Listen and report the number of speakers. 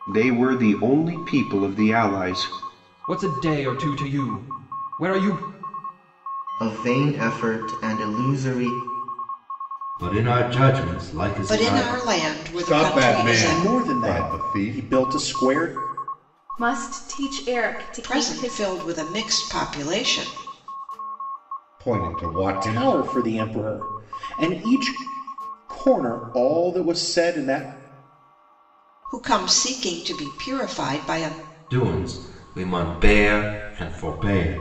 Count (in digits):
8